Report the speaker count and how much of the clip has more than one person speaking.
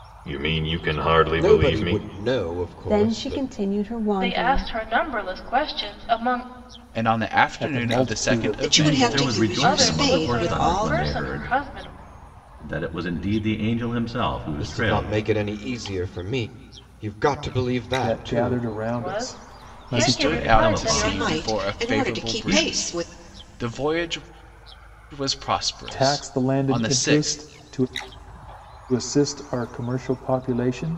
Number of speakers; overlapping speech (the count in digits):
8, about 42%